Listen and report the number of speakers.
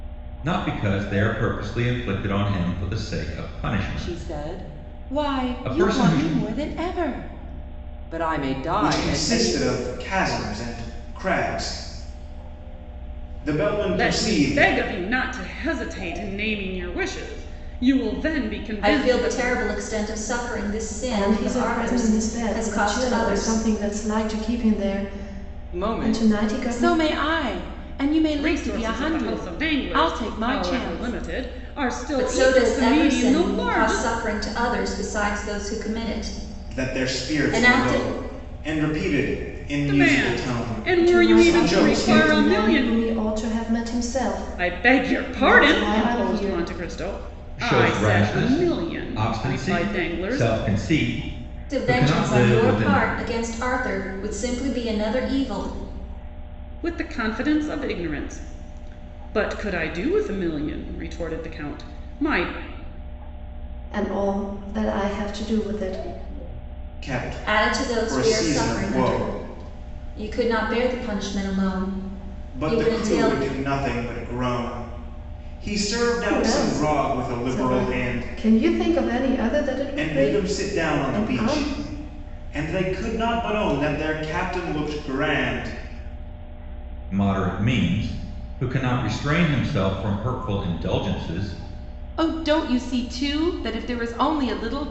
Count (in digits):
6